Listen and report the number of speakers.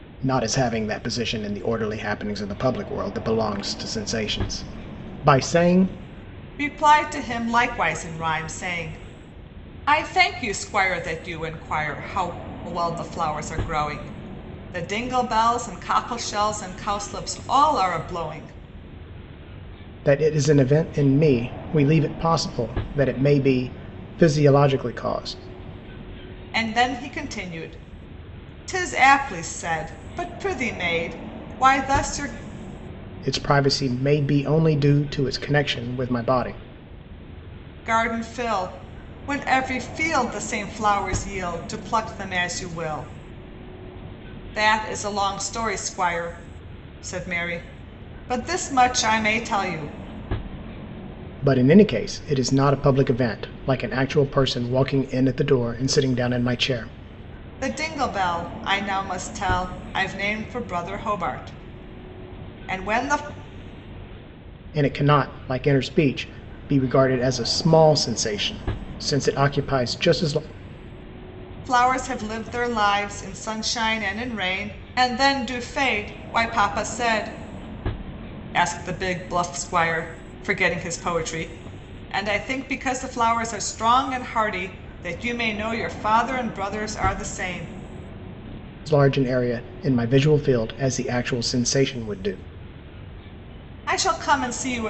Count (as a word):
two